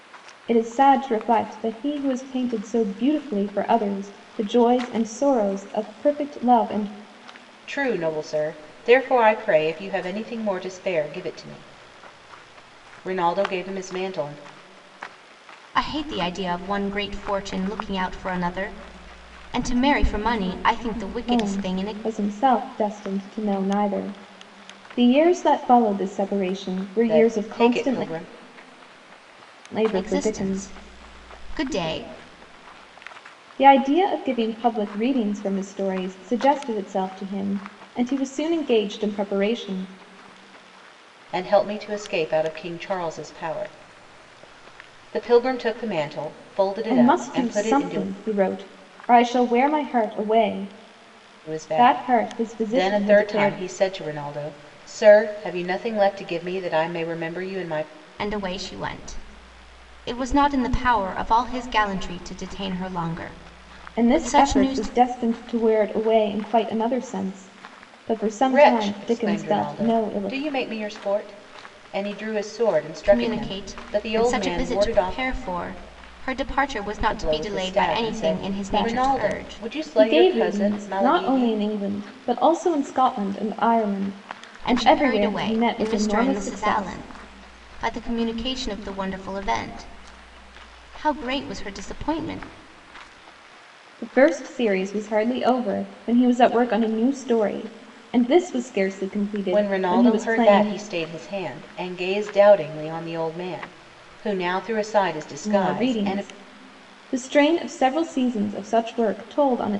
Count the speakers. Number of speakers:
3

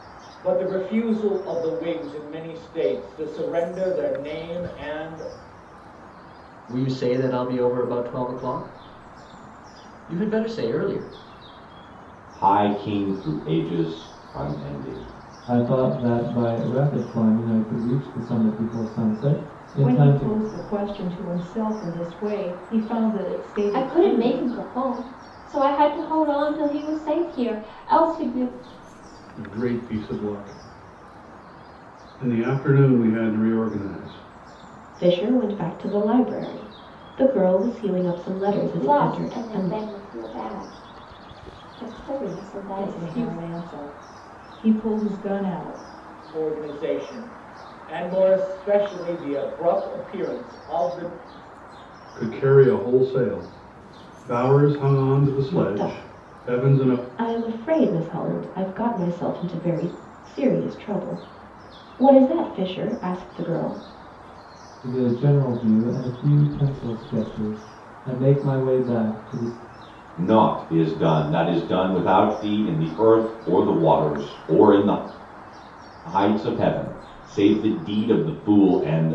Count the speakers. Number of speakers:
8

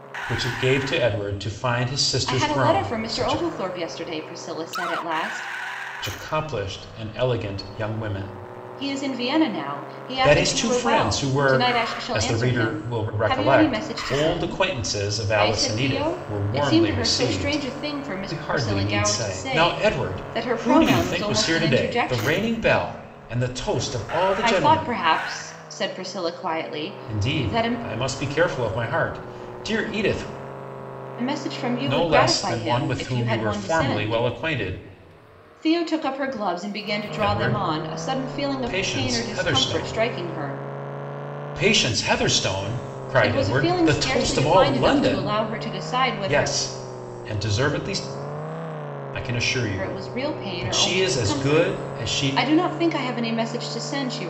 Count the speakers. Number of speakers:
2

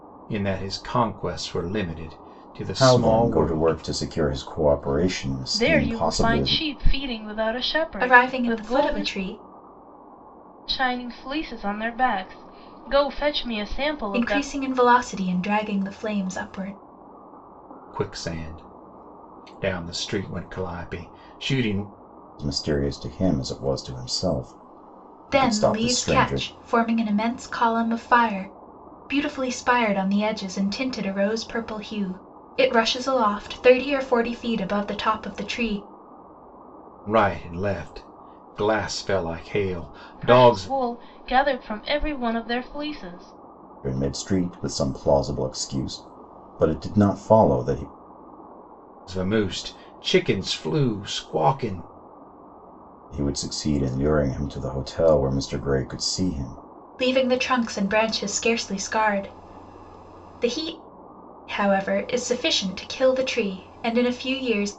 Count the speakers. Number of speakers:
4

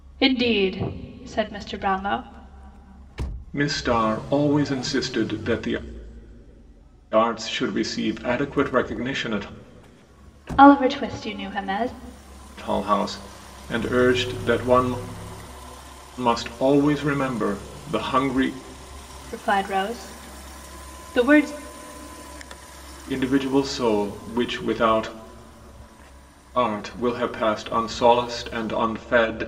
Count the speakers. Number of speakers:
2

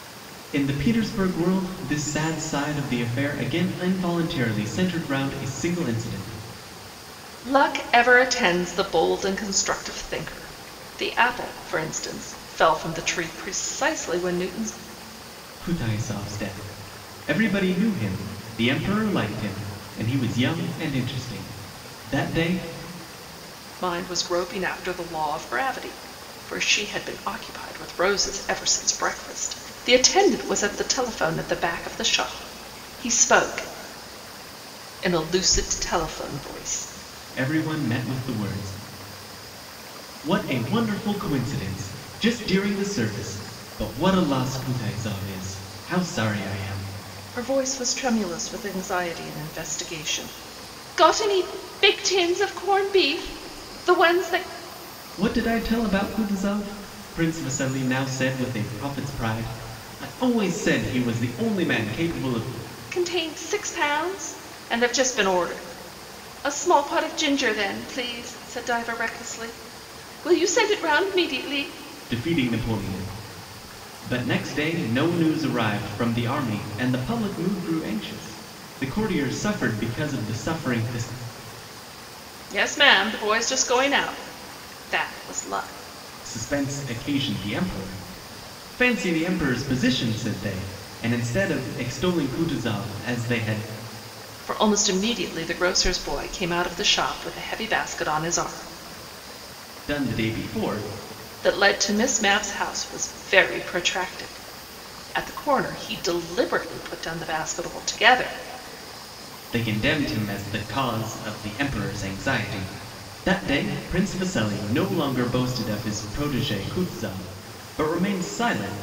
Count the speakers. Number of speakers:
2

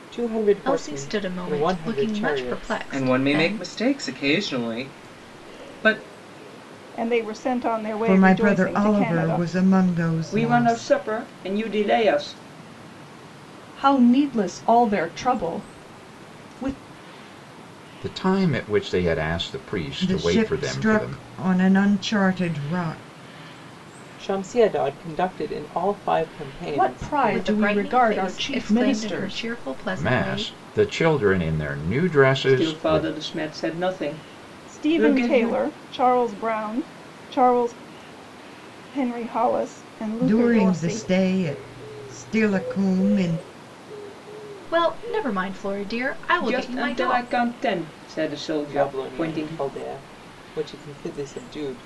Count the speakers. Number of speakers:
8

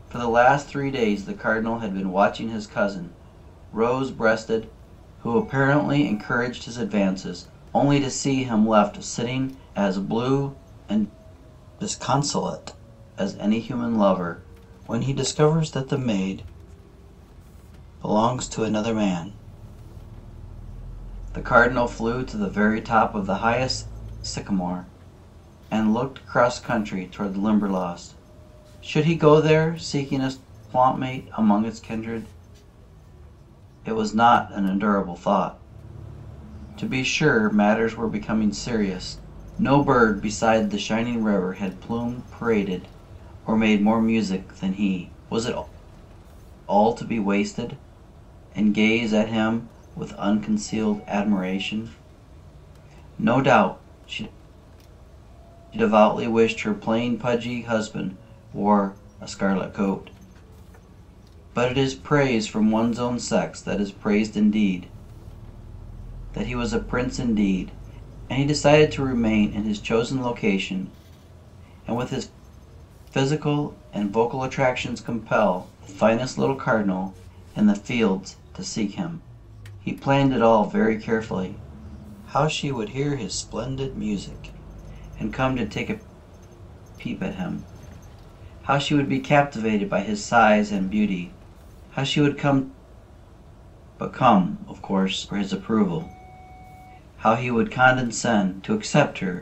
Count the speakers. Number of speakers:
1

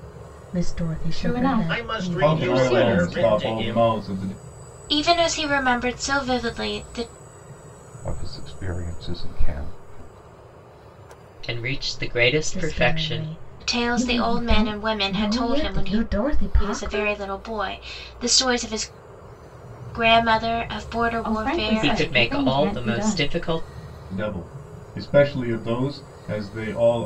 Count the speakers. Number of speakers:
7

